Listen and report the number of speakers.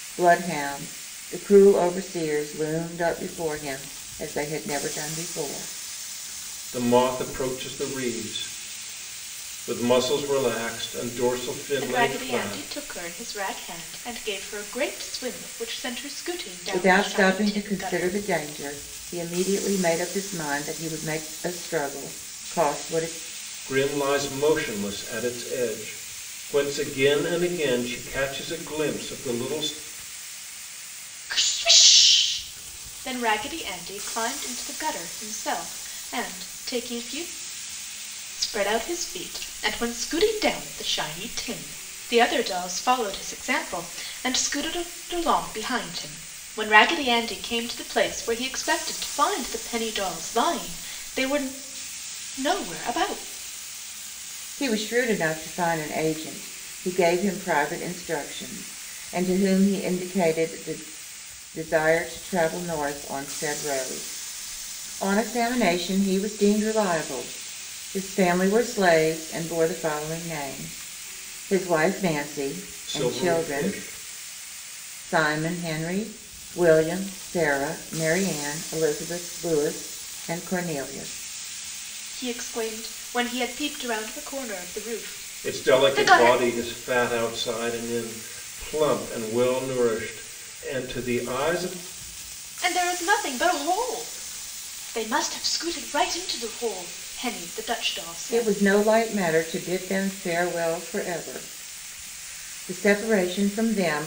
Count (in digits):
3